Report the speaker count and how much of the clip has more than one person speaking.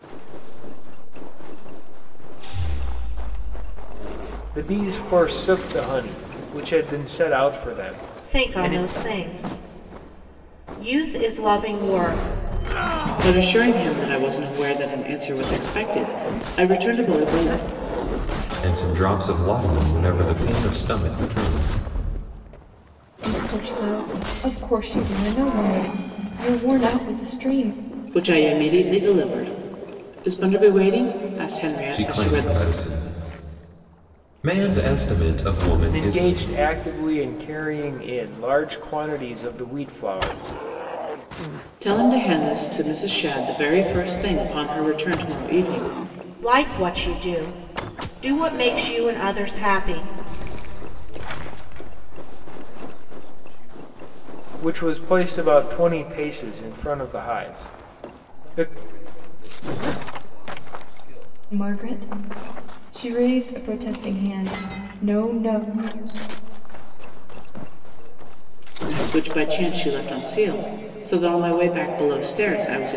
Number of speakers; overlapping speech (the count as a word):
six, about 8%